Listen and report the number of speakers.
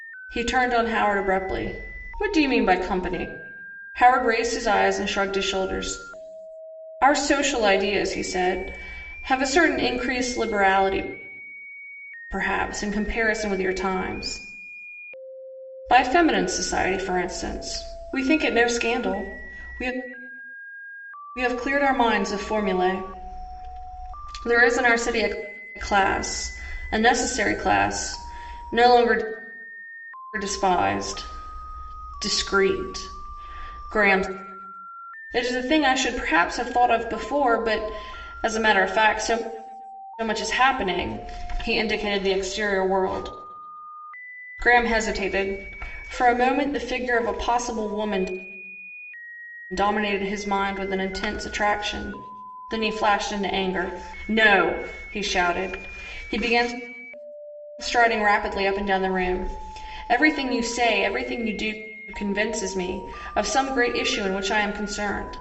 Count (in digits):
1